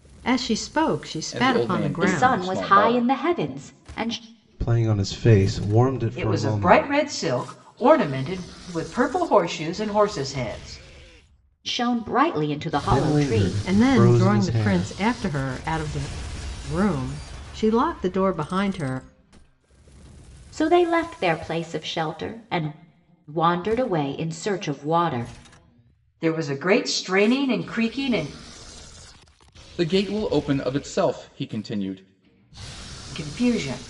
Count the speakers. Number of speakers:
5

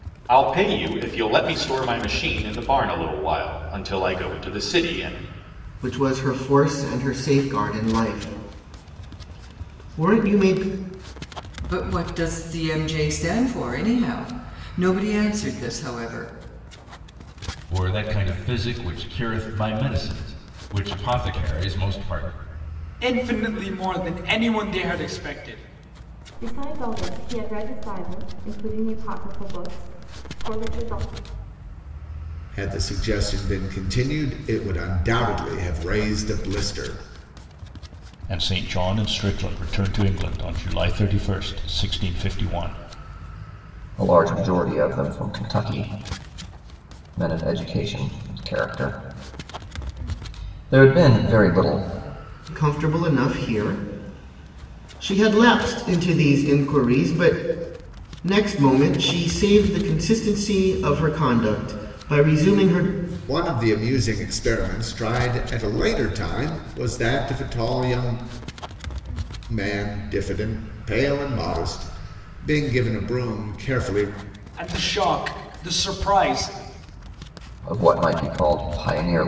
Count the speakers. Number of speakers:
9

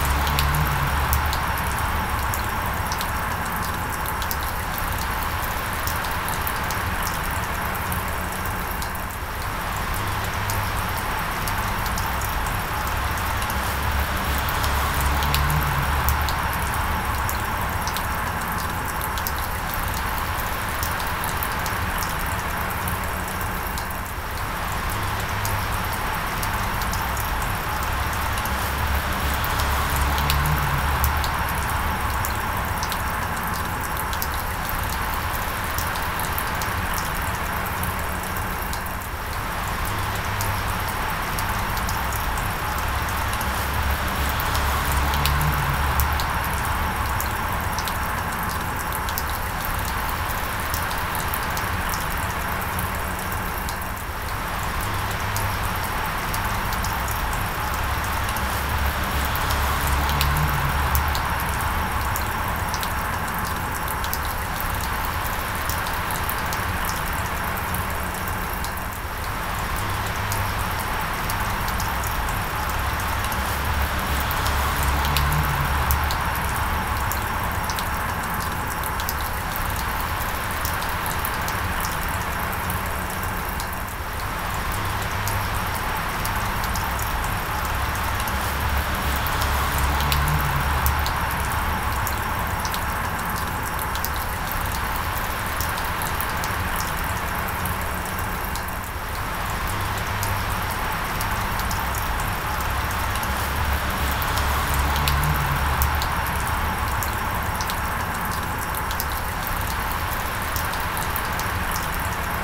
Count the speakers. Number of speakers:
0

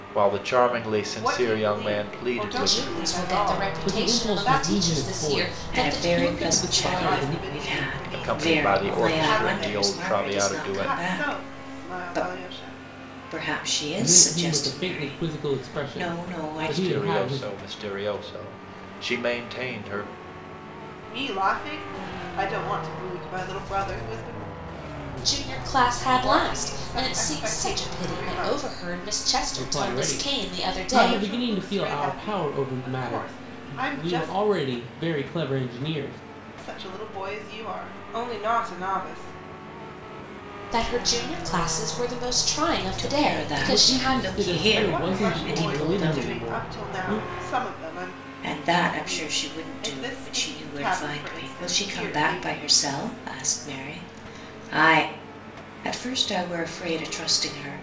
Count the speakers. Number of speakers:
5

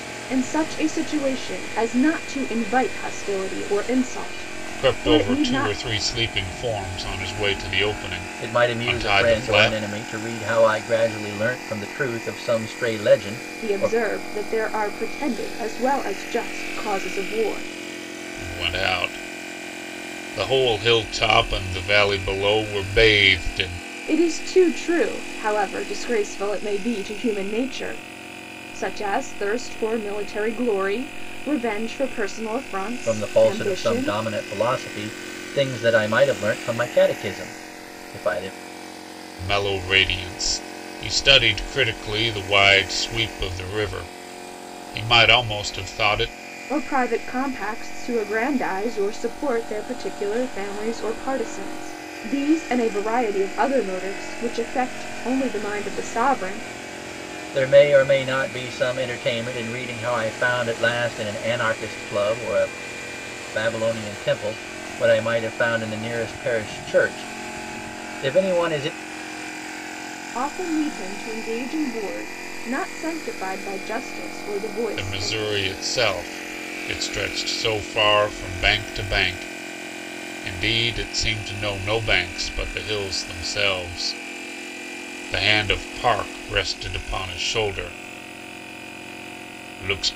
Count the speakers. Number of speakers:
3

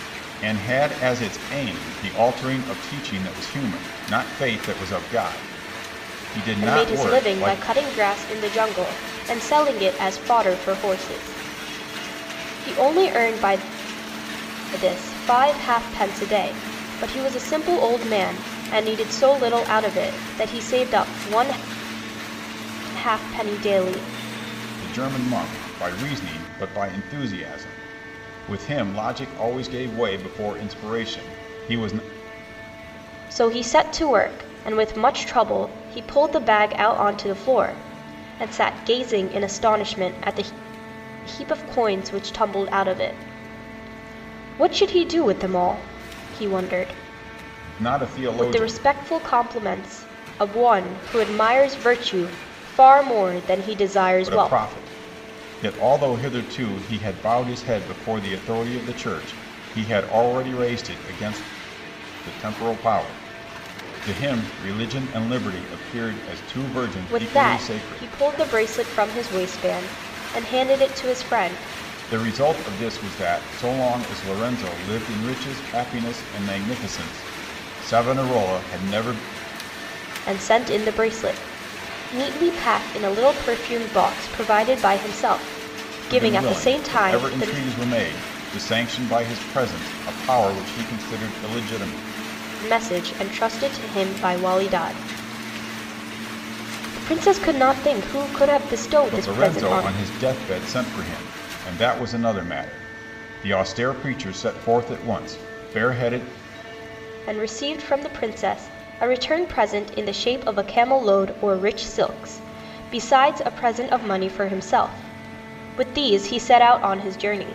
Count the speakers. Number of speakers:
2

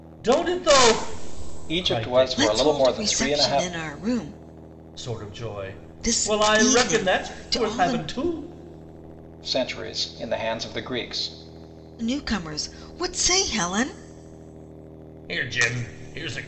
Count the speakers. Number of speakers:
3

